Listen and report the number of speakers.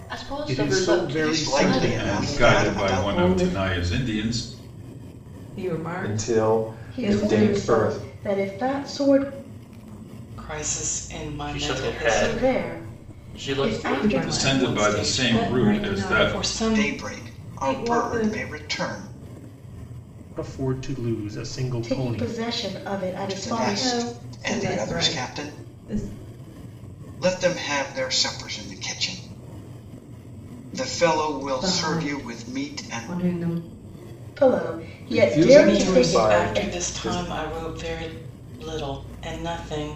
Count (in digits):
10